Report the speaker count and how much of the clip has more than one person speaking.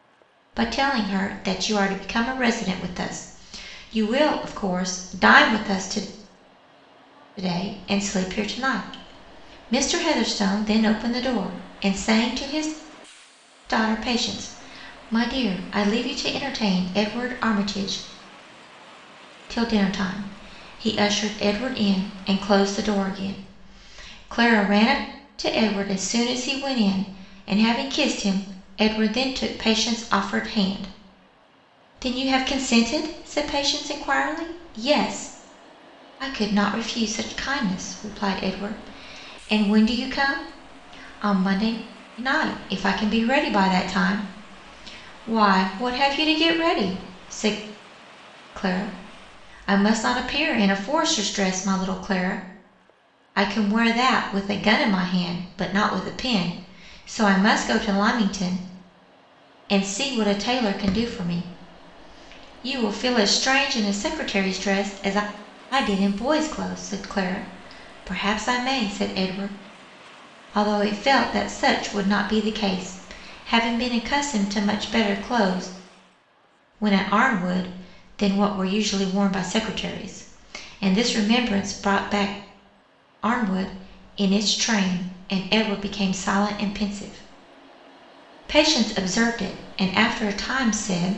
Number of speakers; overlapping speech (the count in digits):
1, no overlap